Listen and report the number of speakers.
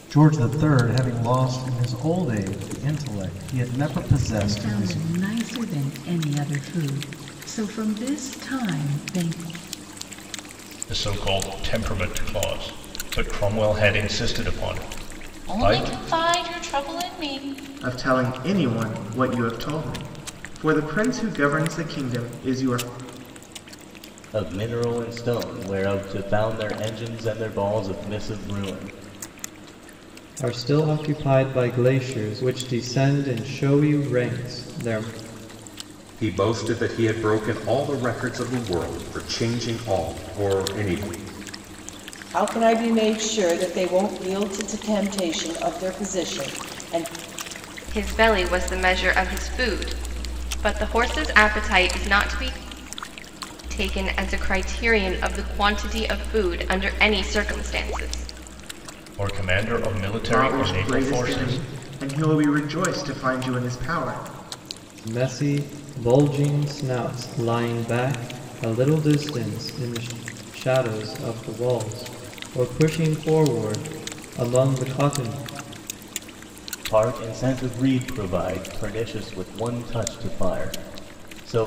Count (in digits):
10